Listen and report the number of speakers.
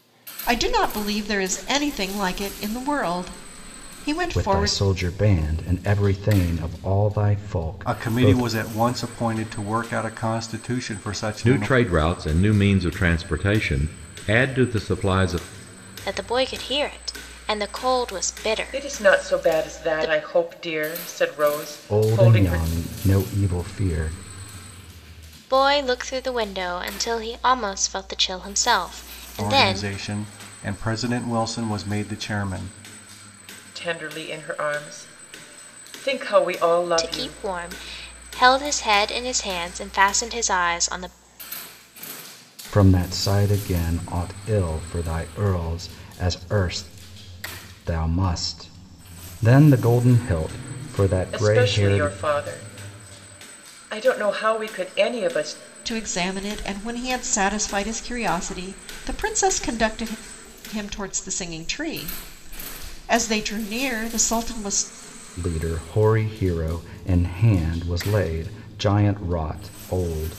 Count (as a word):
six